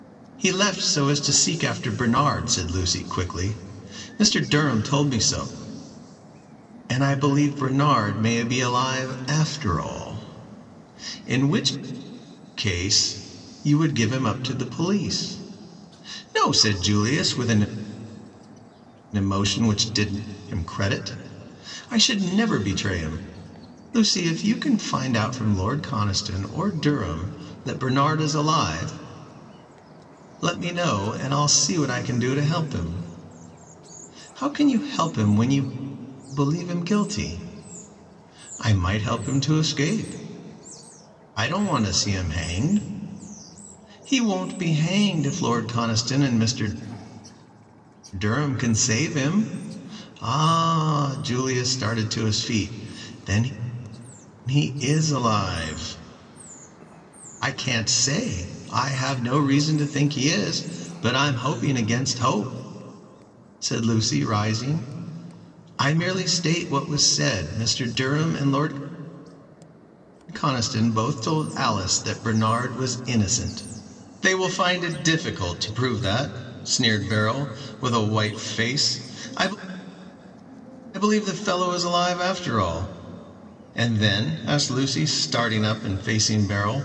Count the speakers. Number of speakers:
1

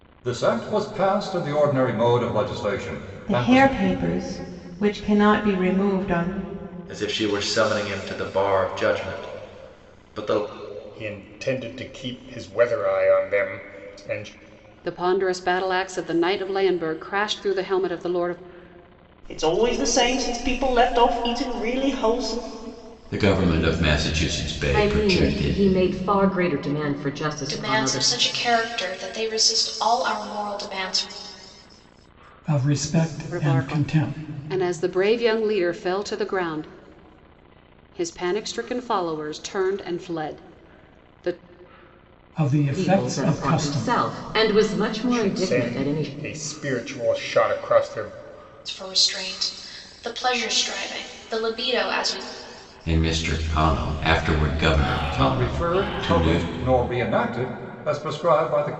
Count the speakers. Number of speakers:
10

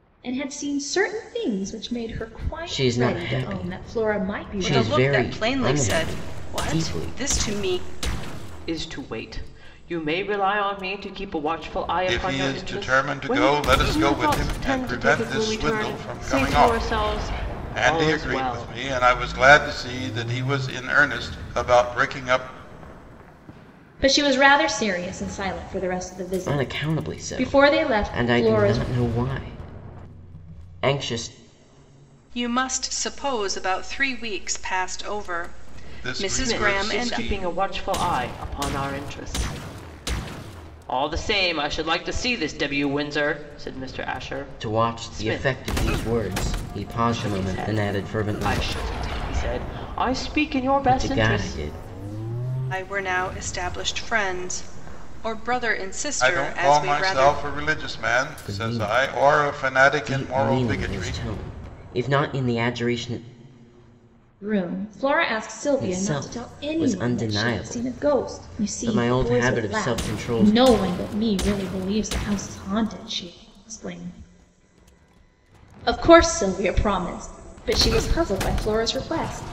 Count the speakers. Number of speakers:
5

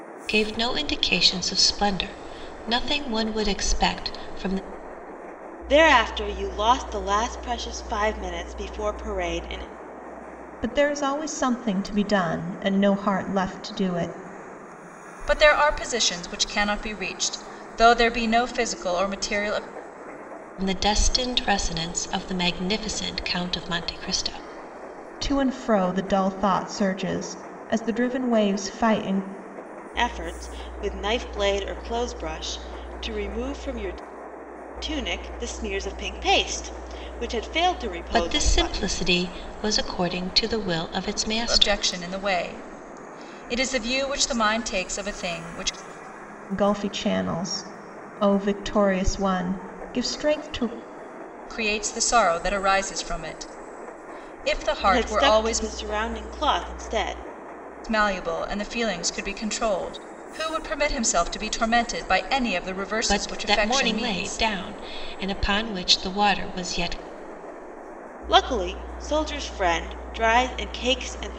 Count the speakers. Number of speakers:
4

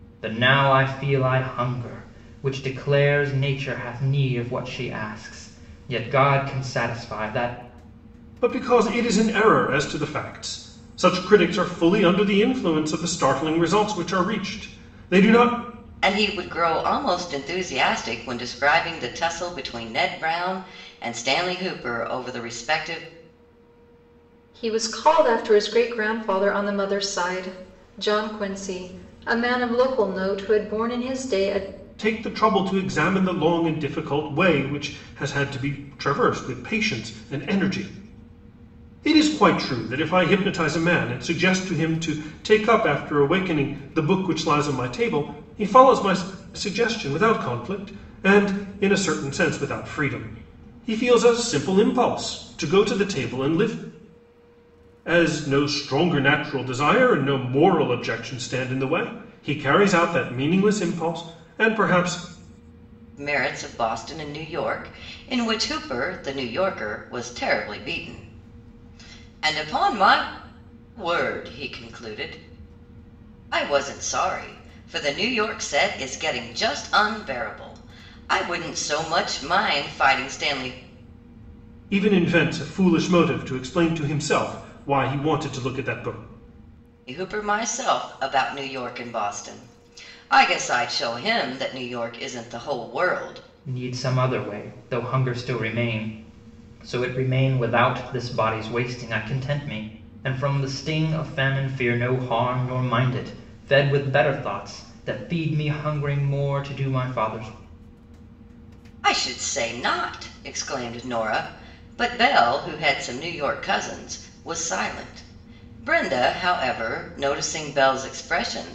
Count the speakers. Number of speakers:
4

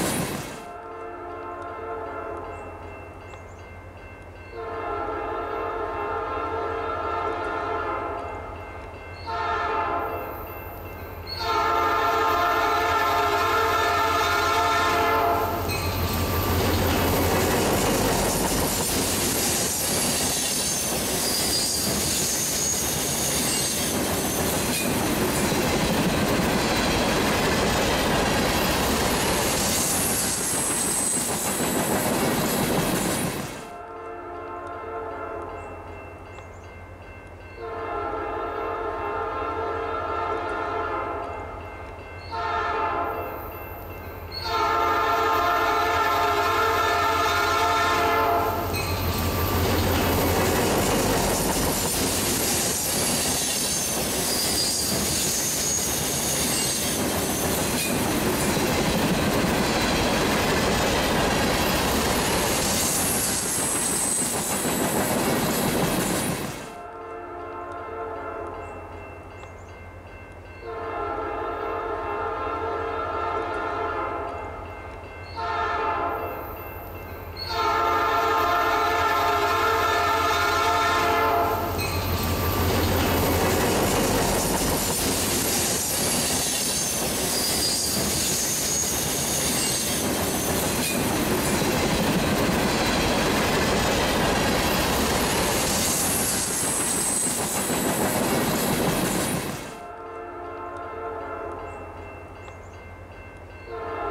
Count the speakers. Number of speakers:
0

